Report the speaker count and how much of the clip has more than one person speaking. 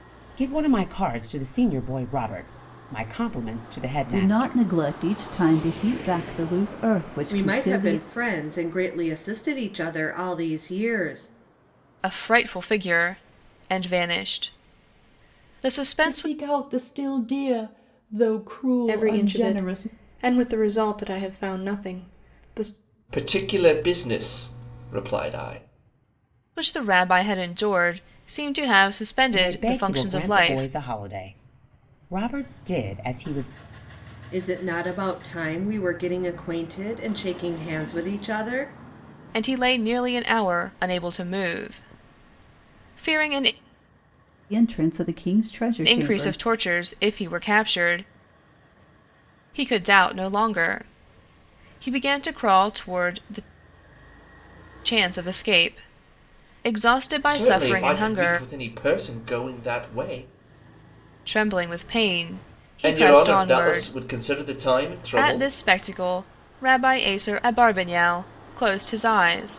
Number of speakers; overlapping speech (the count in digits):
7, about 11%